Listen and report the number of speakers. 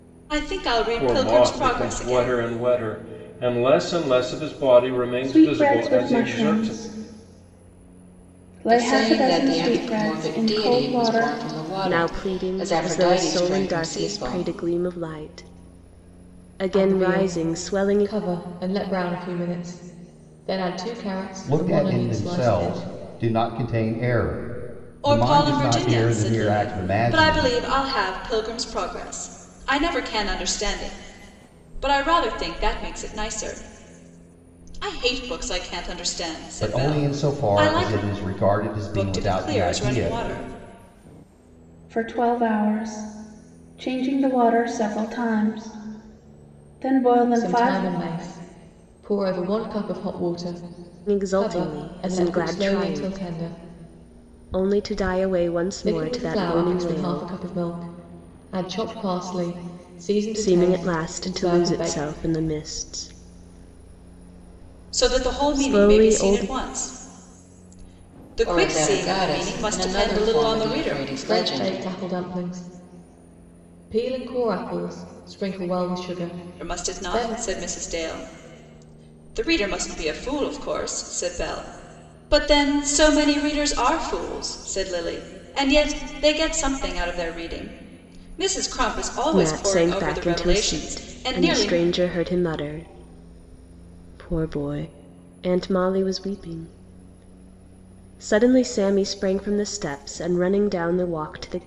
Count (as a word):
seven